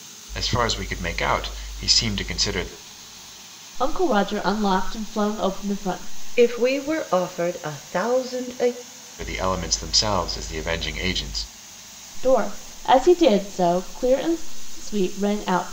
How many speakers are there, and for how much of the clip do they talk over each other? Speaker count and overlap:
3, no overlap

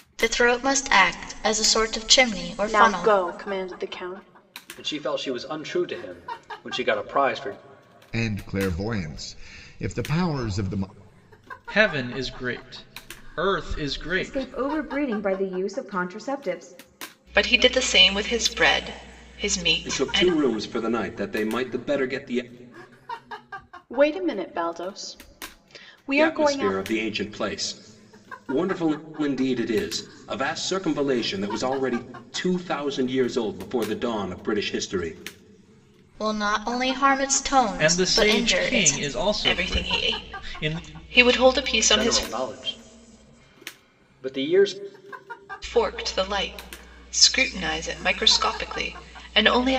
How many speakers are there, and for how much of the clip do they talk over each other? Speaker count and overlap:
8, about 10%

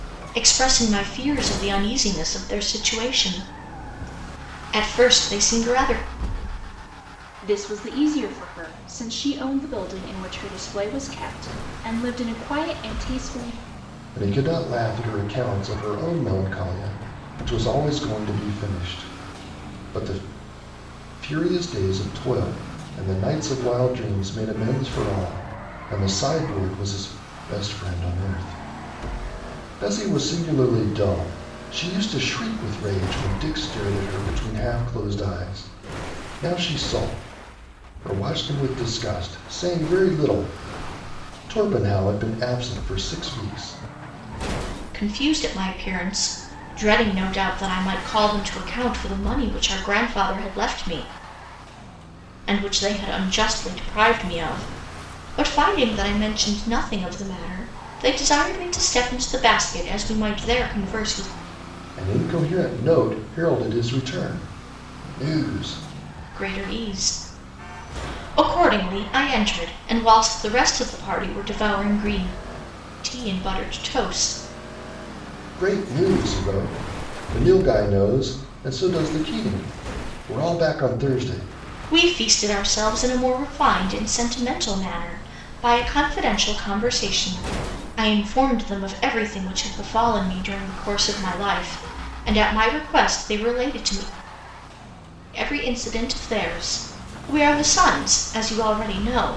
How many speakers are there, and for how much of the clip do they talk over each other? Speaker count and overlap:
3, no overlap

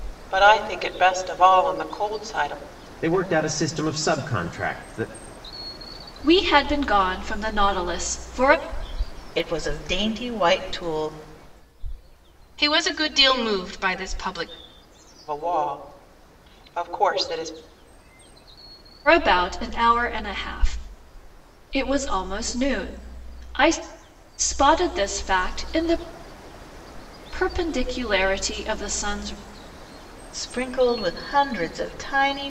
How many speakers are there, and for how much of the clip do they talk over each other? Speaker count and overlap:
5, no overlap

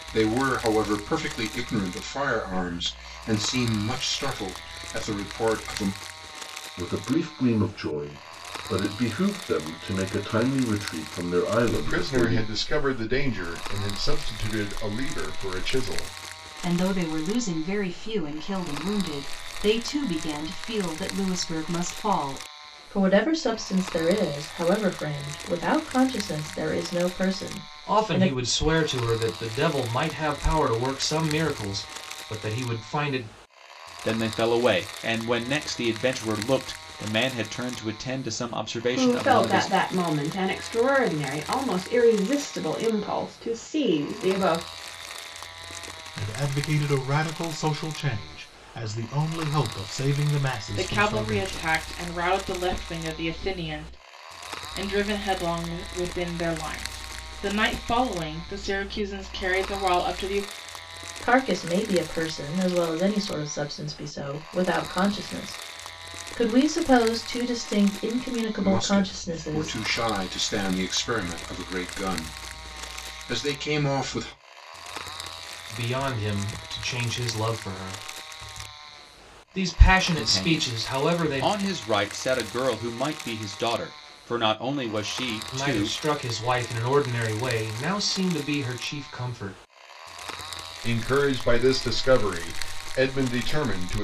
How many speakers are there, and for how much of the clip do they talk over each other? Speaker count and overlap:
10, about 7%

